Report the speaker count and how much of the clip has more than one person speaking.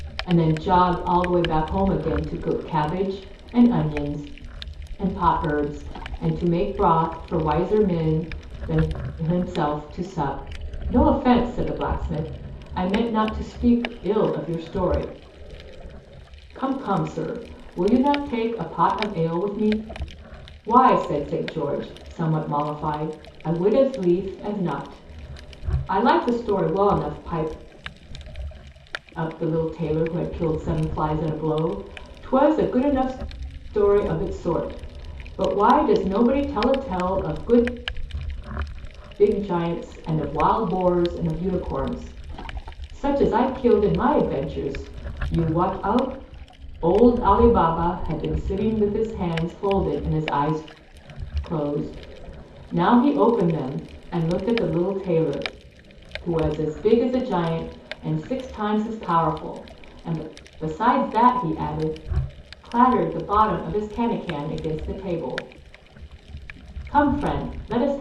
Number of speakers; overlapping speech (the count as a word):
one, no overlap